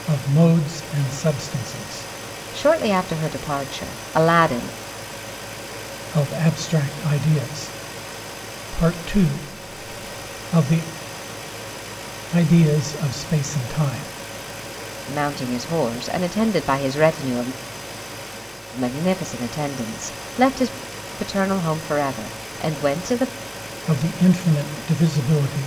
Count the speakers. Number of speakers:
two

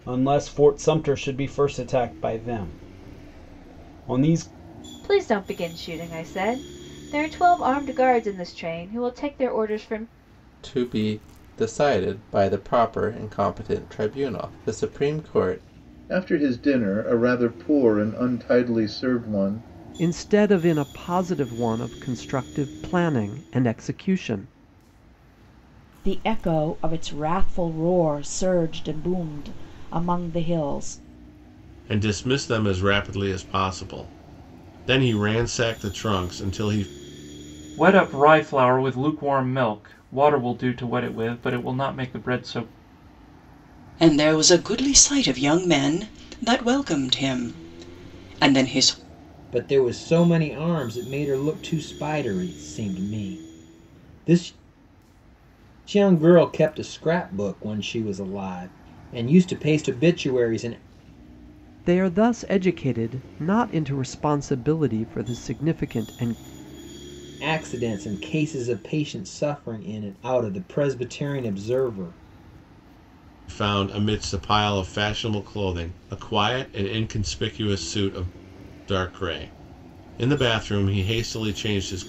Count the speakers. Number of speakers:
ten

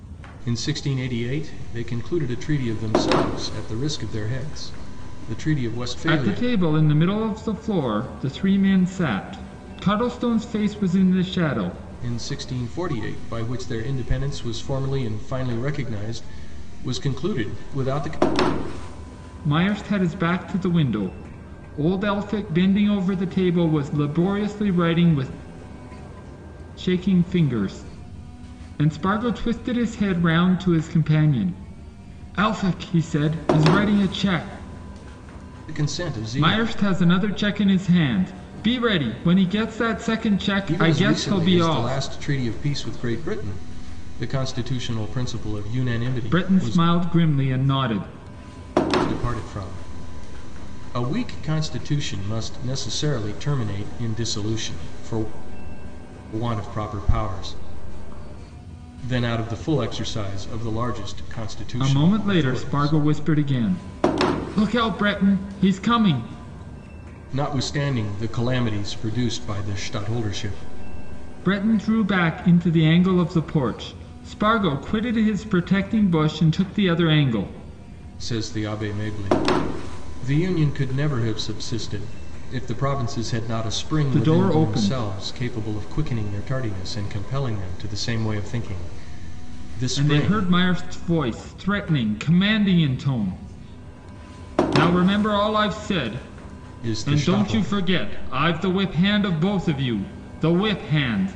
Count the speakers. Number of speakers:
two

